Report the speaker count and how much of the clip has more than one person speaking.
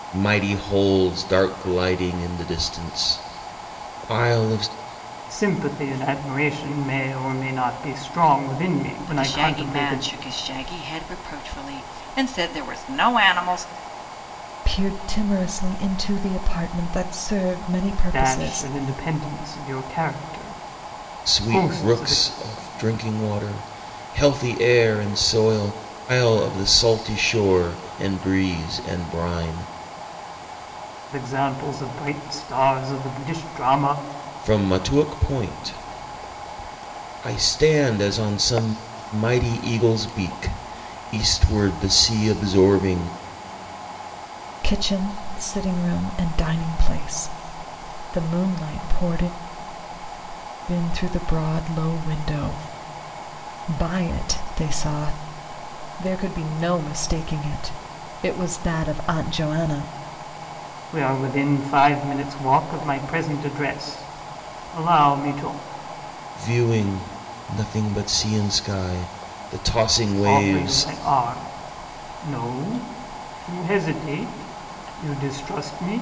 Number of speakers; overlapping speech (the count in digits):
4, about 4%